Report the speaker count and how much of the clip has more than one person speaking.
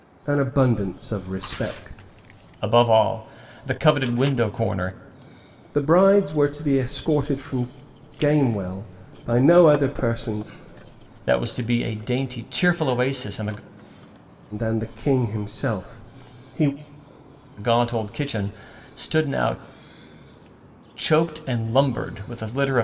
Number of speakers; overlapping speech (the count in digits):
2, no overlap